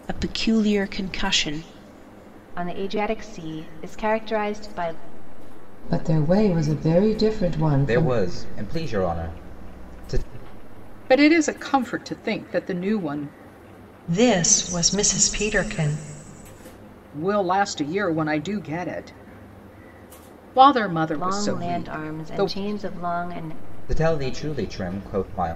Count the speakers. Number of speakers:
six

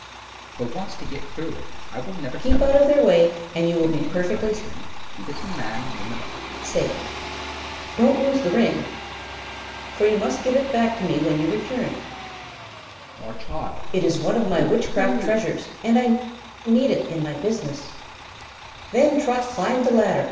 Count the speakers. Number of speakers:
two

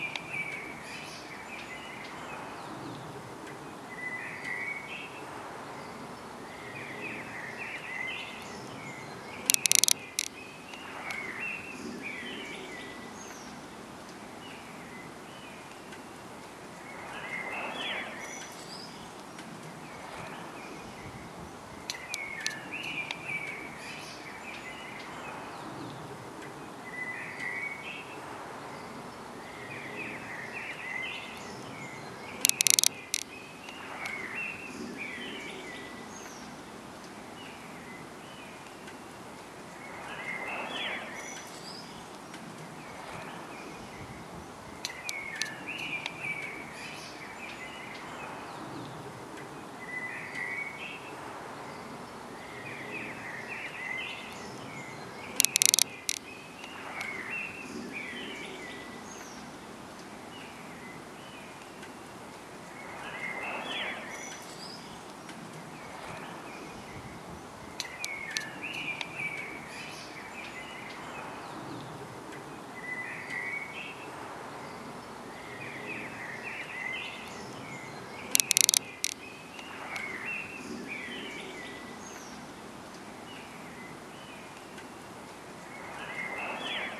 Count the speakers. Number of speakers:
zero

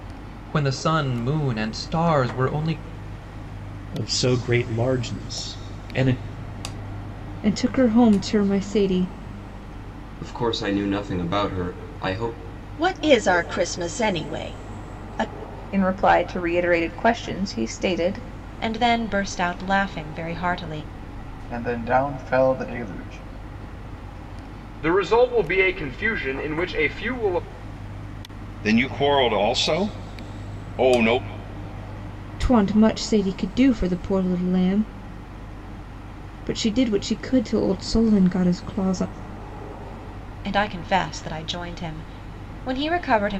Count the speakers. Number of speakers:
ten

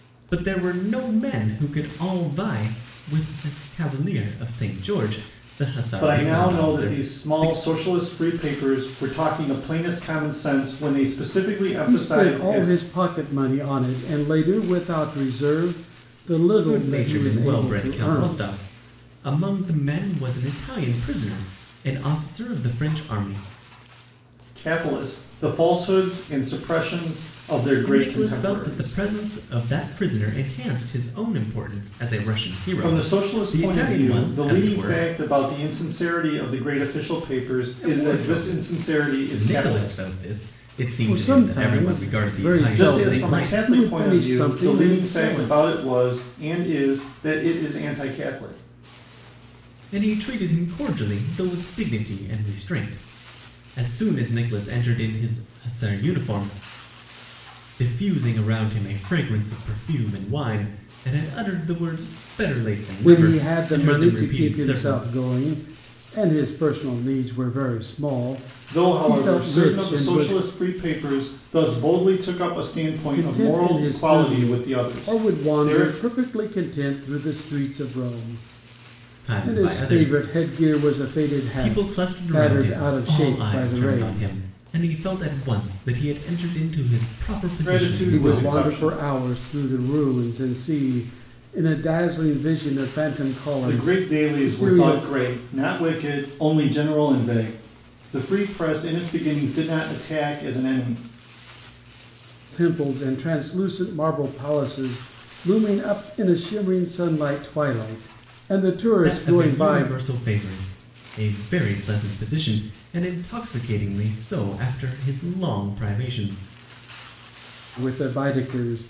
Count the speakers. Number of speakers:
three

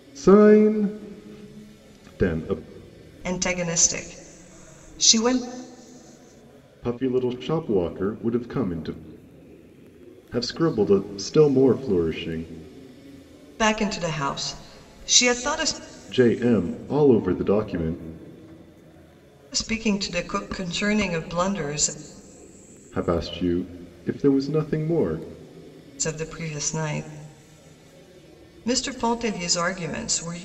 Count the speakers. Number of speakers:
two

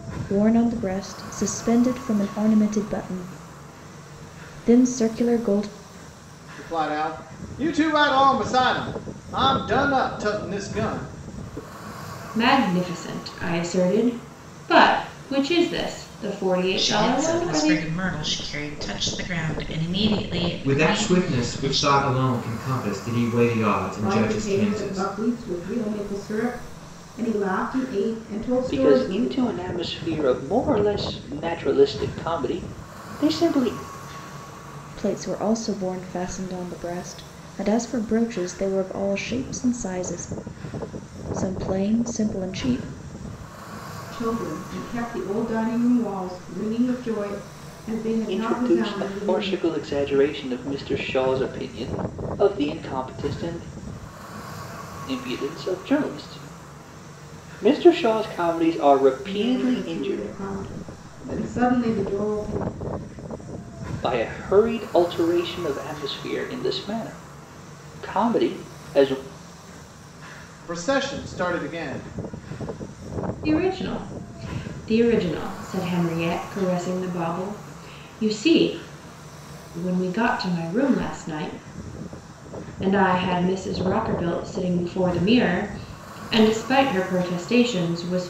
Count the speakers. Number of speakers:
seven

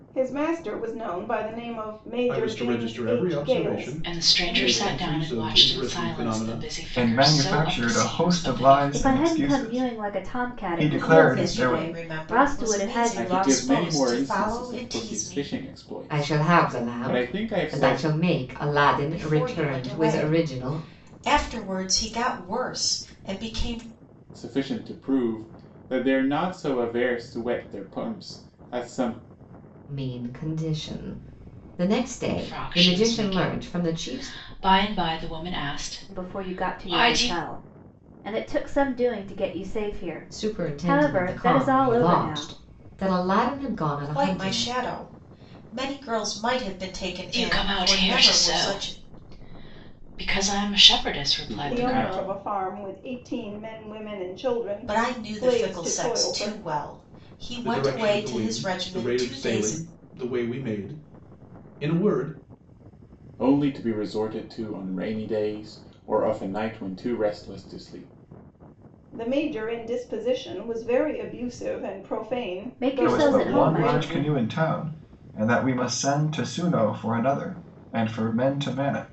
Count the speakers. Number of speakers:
eight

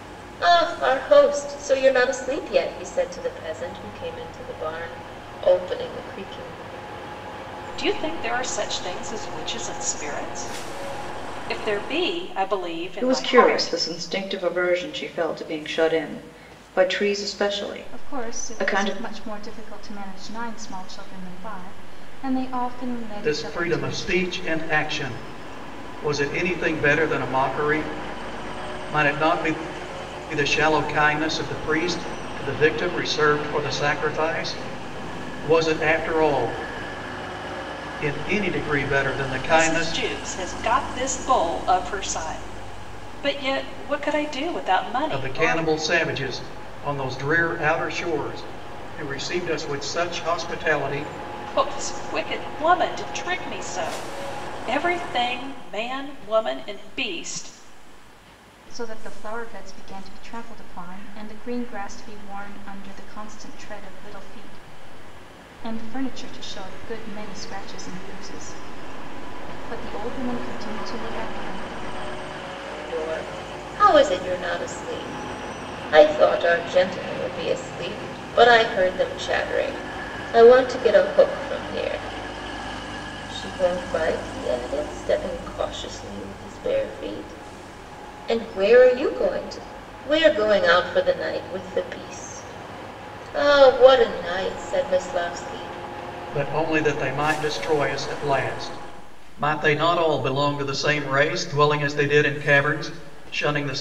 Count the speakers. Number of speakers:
five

